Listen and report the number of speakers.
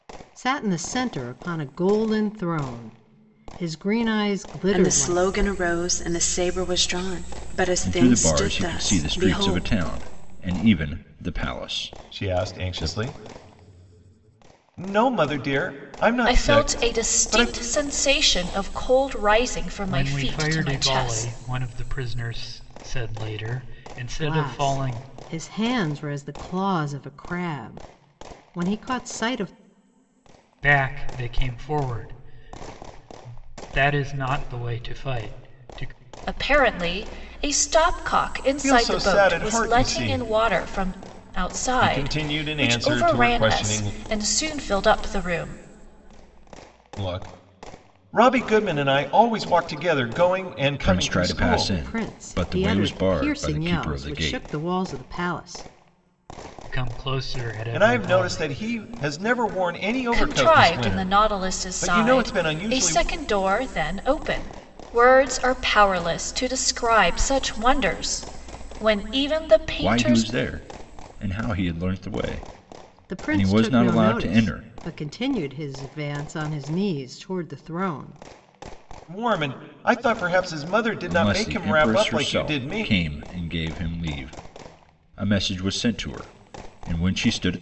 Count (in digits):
6